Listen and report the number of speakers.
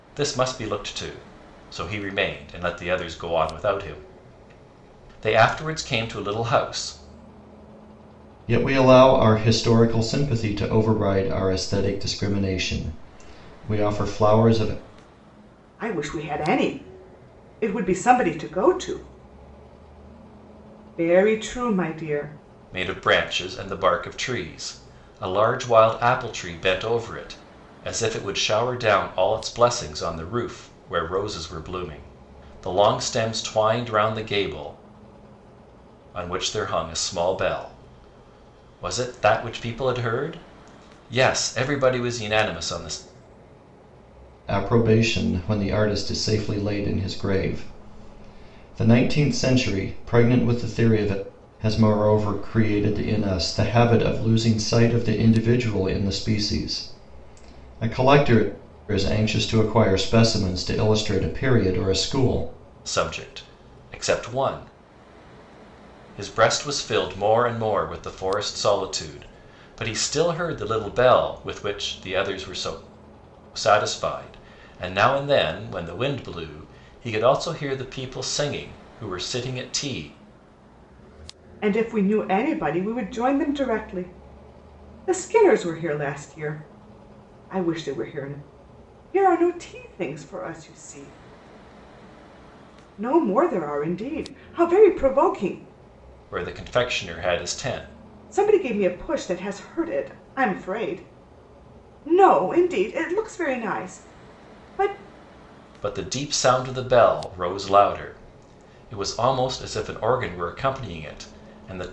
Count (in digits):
3